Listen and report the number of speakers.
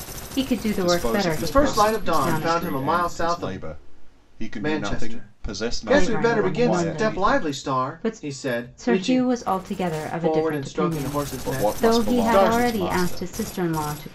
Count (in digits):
3